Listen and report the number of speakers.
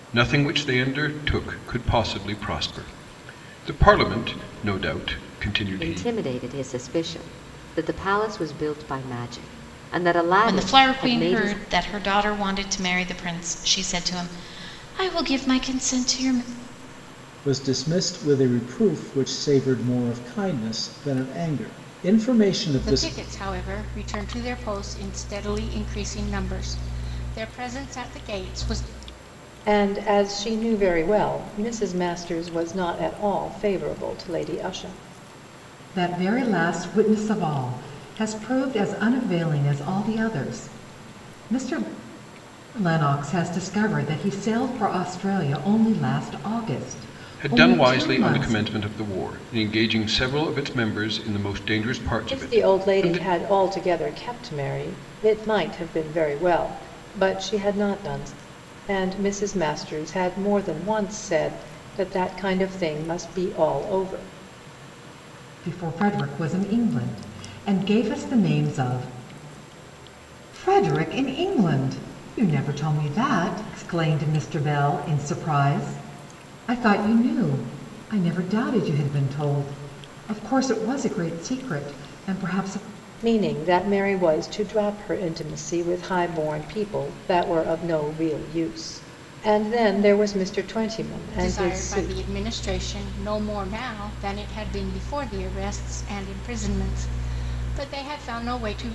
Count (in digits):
7